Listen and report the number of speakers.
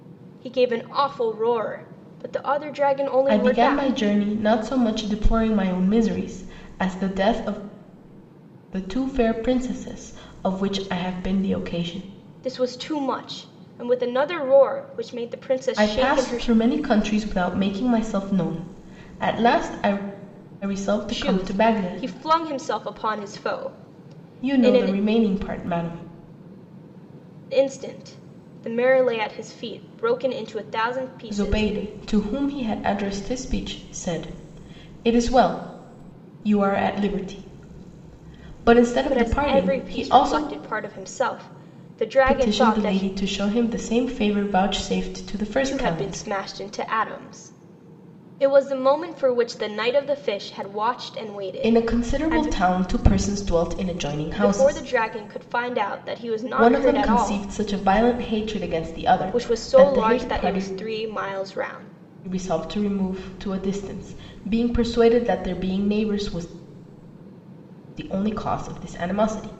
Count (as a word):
two